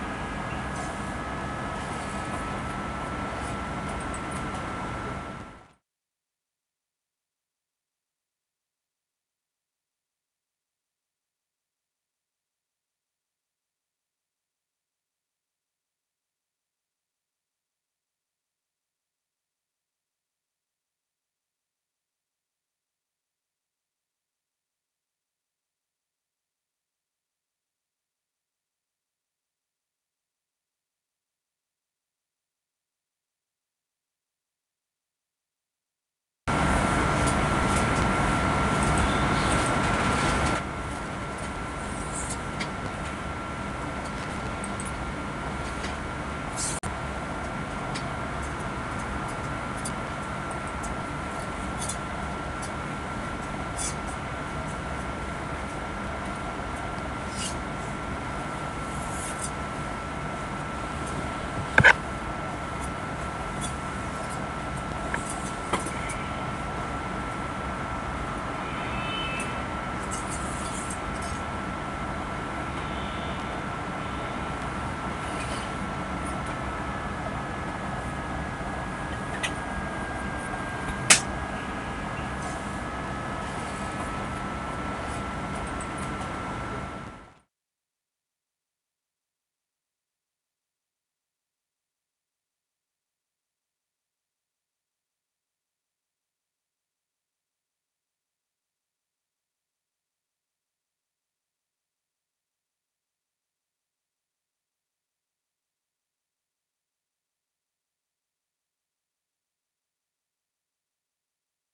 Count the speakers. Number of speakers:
0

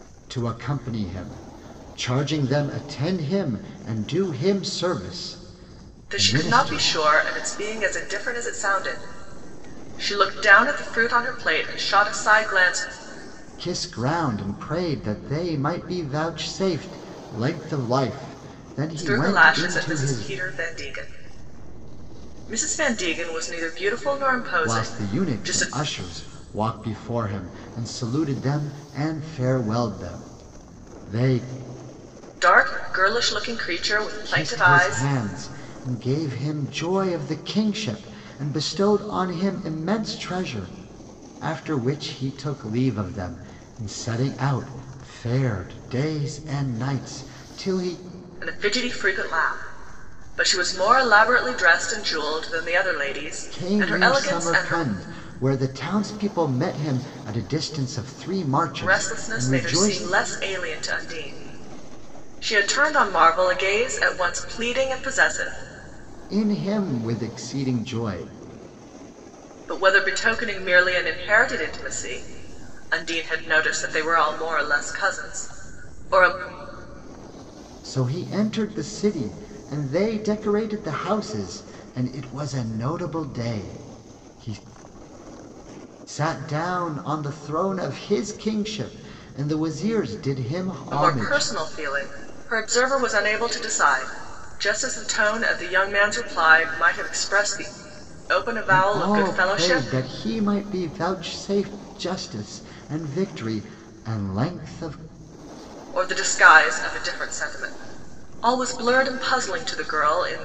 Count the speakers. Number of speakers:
2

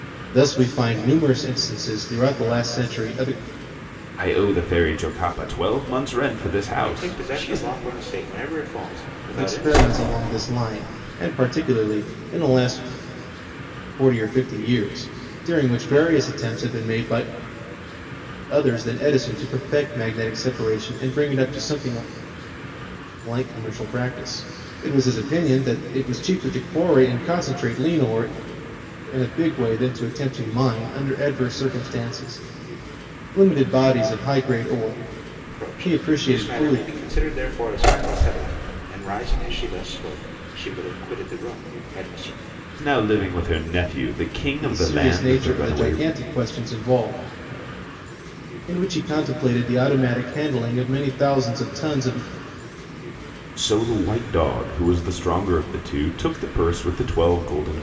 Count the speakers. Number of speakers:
3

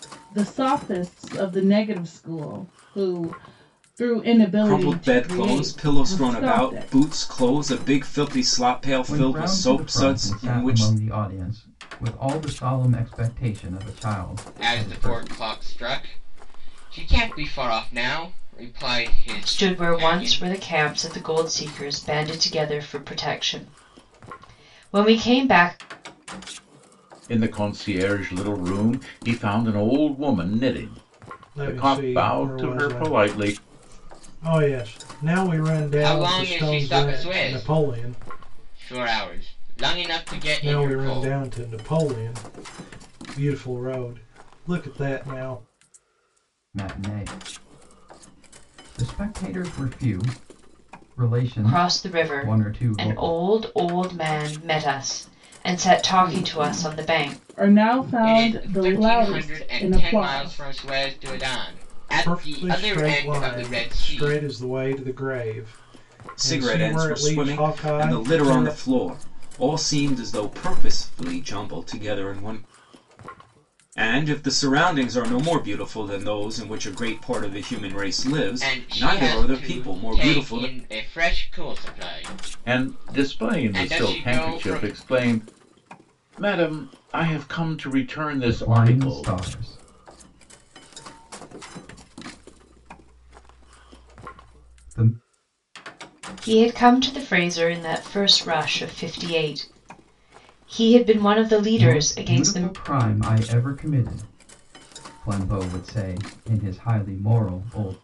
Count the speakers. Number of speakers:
7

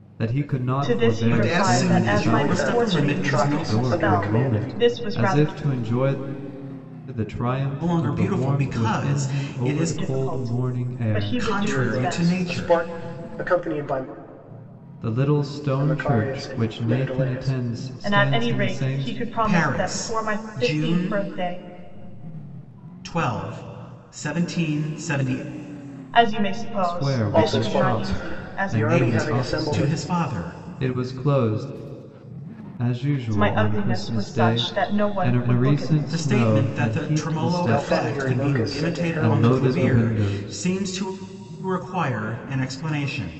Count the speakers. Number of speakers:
4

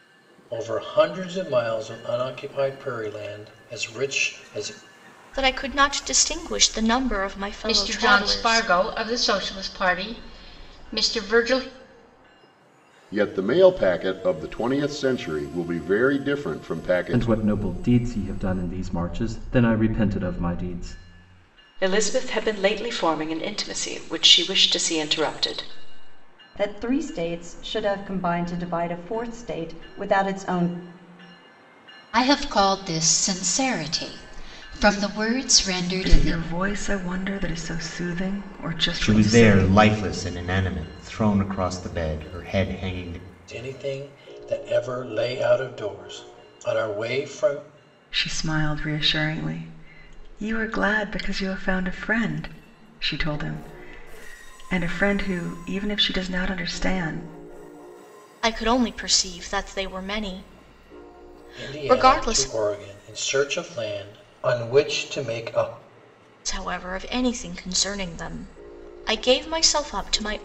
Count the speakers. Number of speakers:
10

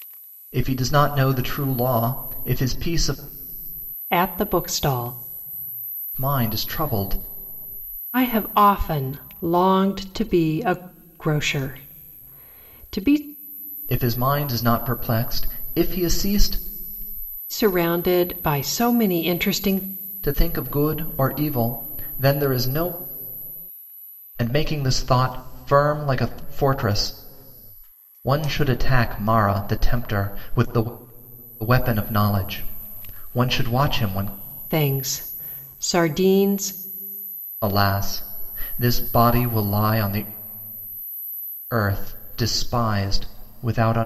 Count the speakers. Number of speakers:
2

